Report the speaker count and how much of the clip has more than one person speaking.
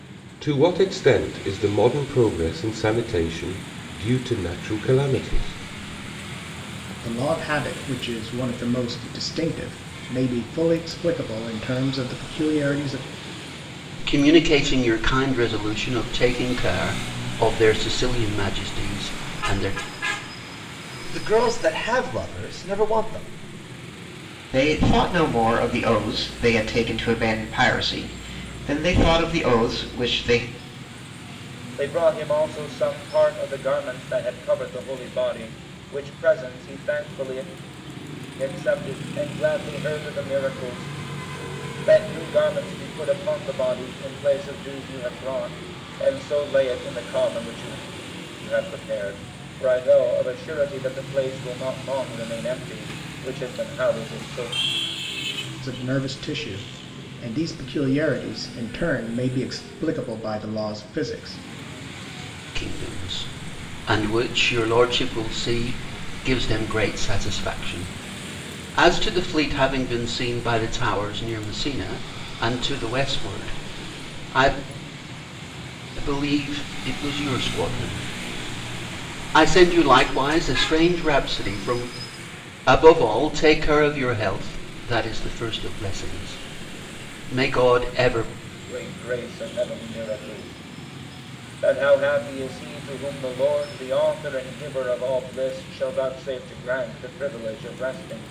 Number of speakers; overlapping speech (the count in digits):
6, no overlap